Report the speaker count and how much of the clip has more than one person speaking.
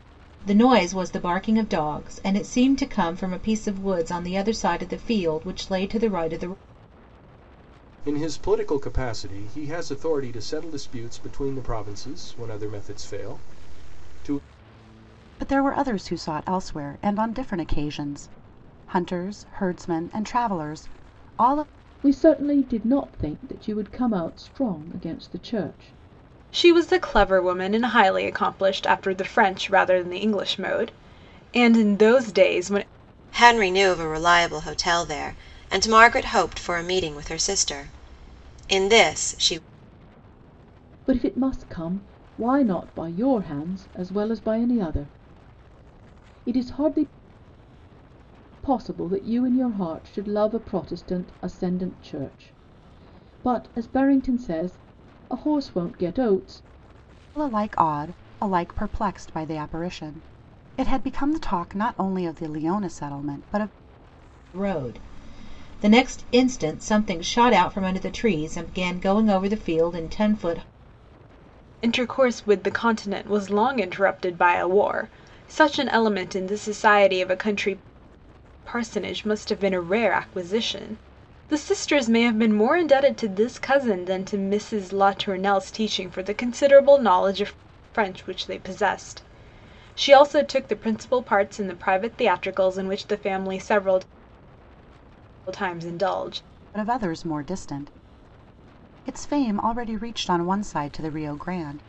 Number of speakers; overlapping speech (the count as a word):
six, no overlap